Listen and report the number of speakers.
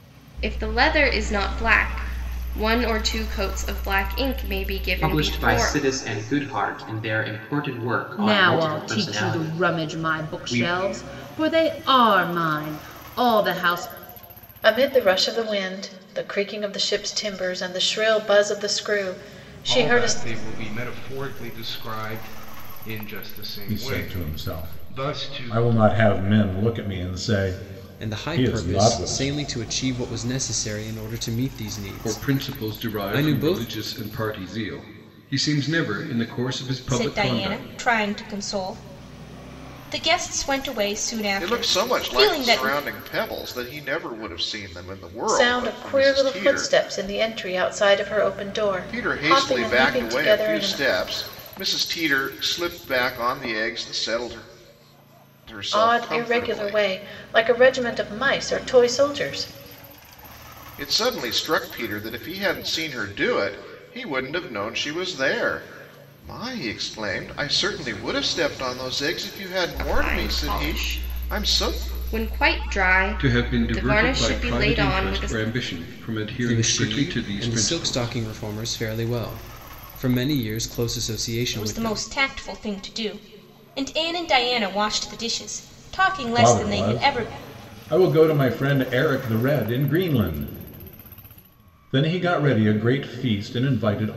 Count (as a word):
ten